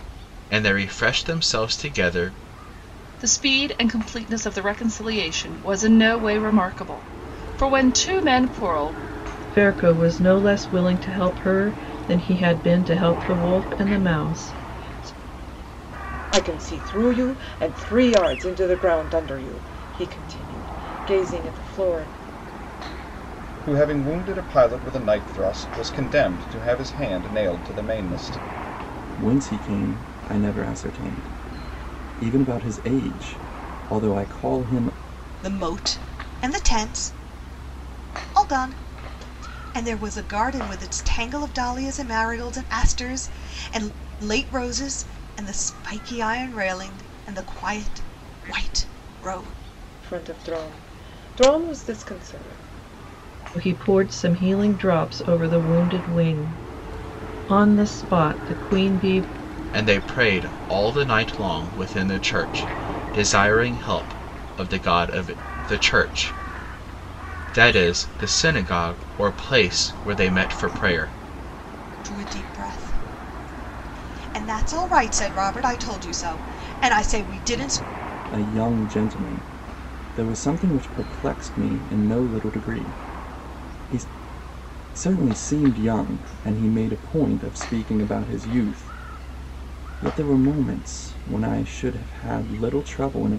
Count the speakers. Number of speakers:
seven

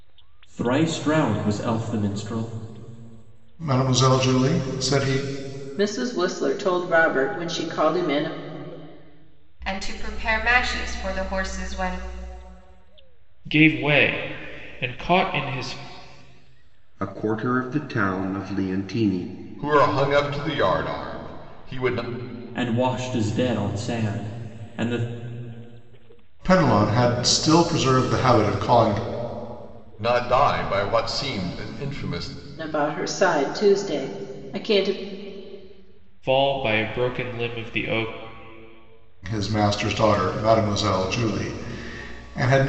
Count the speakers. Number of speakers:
seven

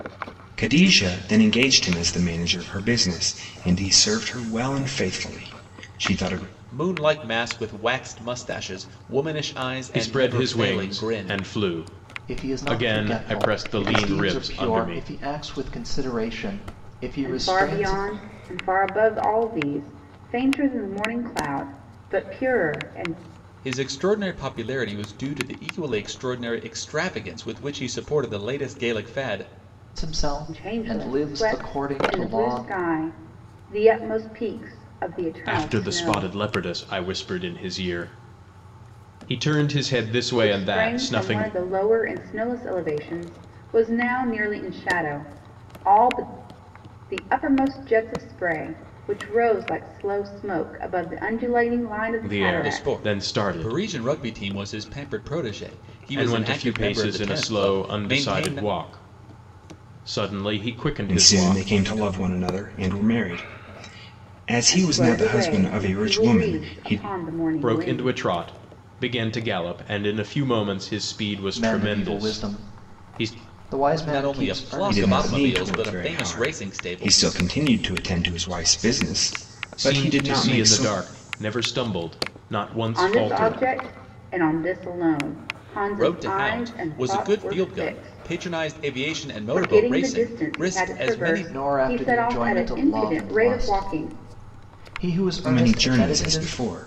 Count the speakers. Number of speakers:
five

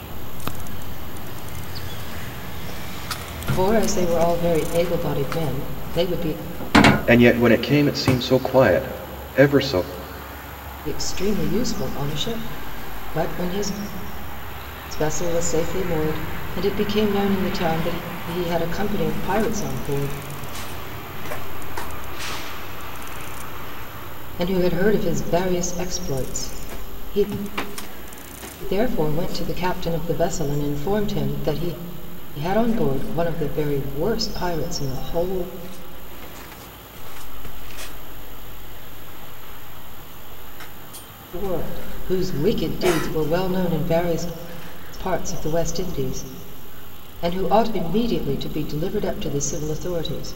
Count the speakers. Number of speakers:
three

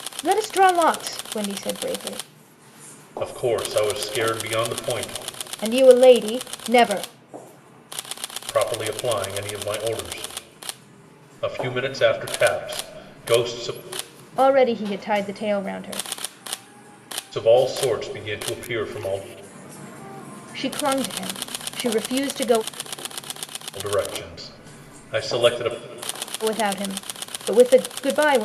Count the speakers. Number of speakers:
two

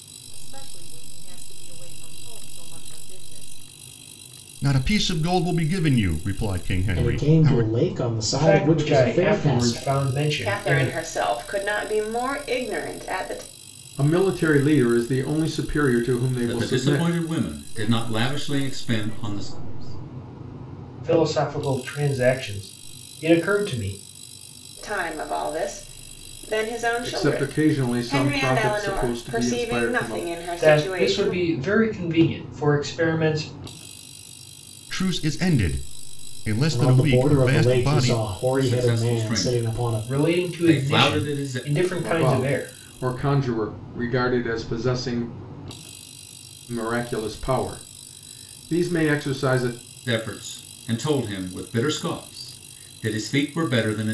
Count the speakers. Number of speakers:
seven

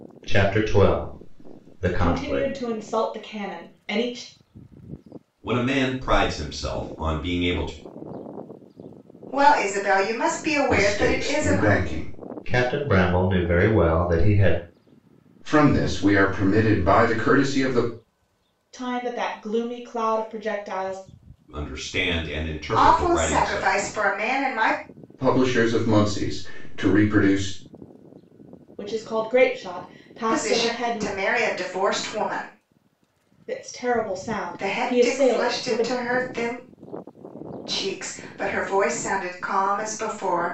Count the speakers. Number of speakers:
five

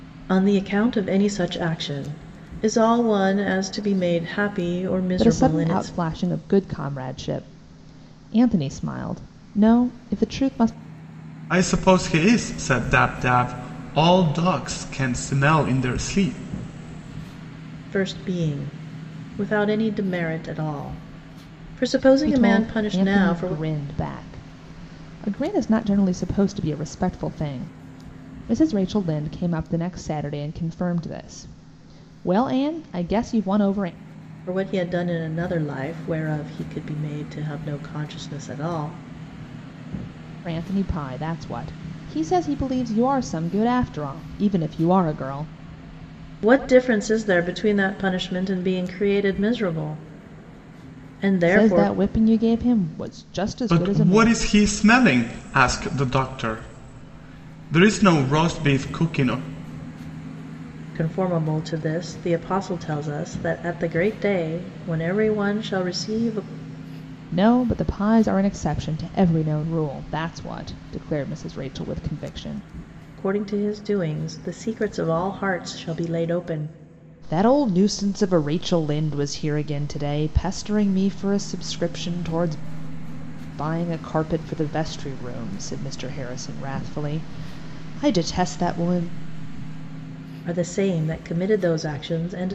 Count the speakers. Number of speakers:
three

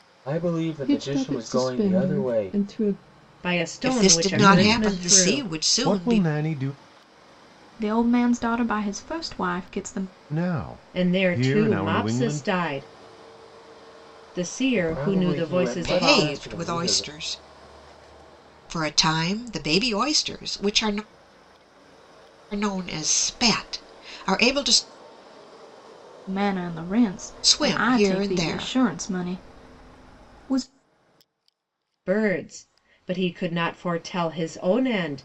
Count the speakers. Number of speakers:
six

